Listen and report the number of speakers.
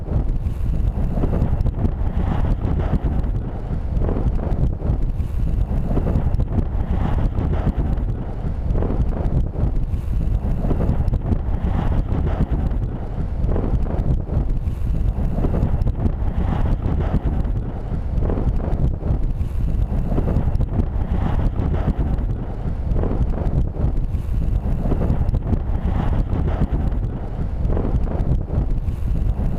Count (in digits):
0